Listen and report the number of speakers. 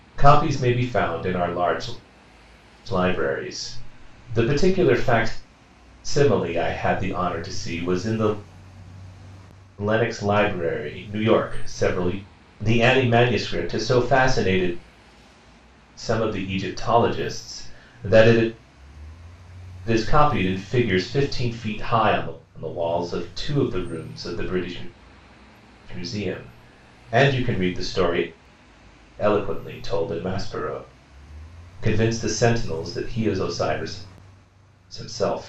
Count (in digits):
1